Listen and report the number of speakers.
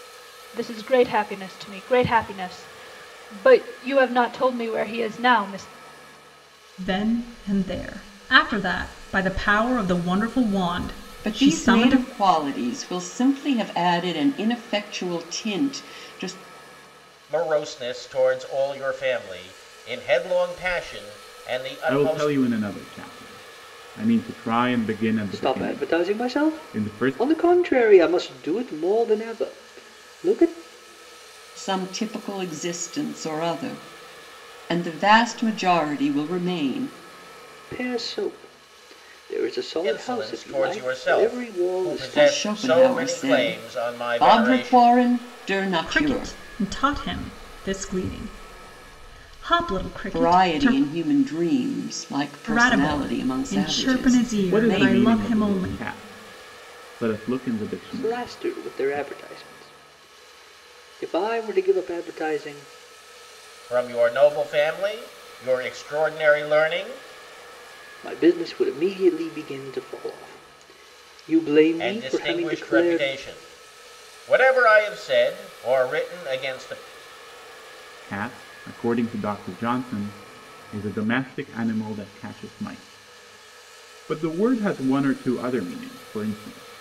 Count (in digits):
6